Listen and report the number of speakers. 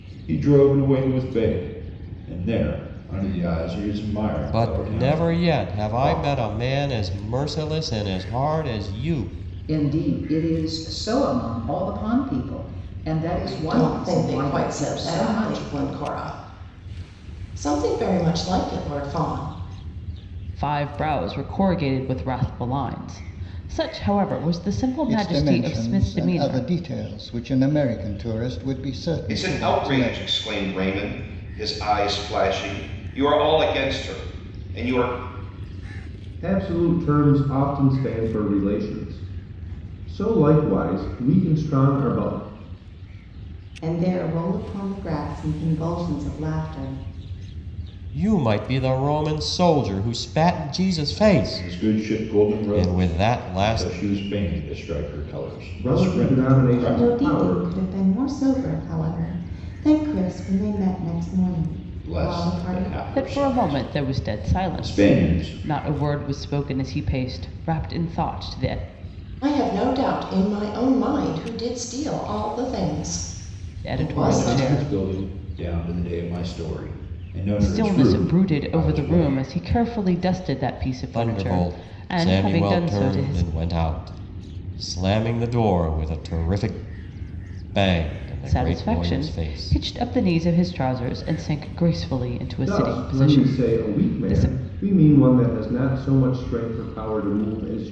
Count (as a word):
nine